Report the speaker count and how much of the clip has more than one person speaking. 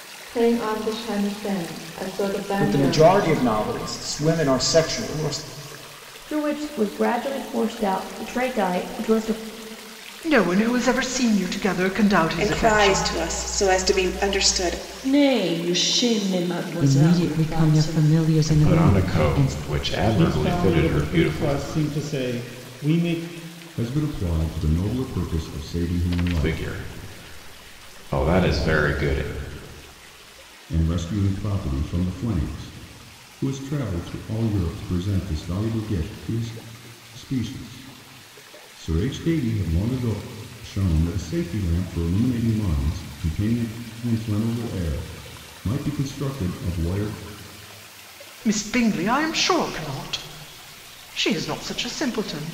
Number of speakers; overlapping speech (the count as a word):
ten, about 11%